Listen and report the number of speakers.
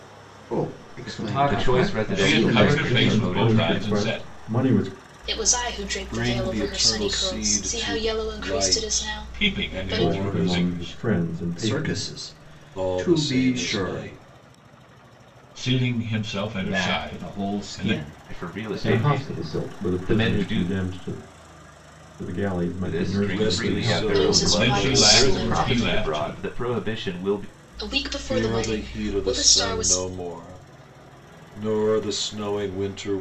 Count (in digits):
7